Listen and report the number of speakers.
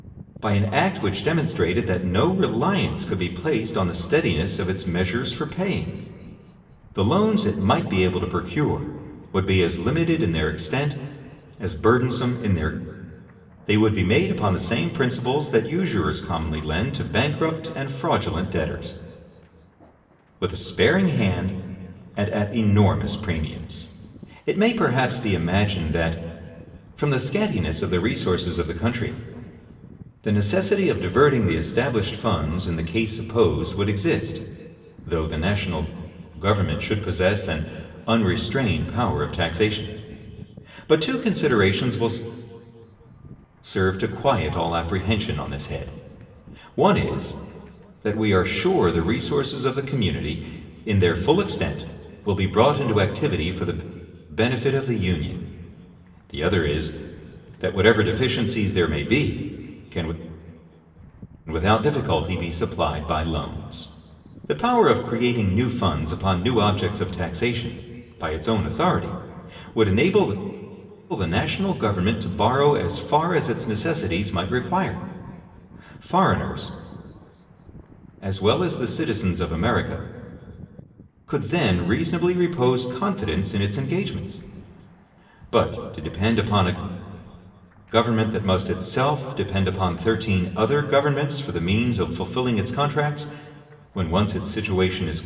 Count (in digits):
1